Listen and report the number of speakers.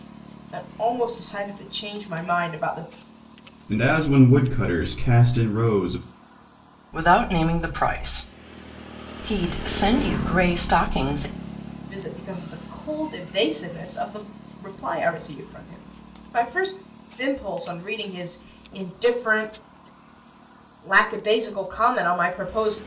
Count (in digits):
3